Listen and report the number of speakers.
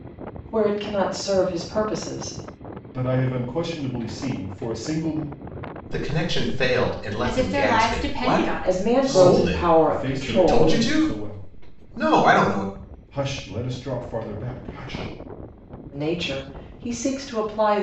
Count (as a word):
four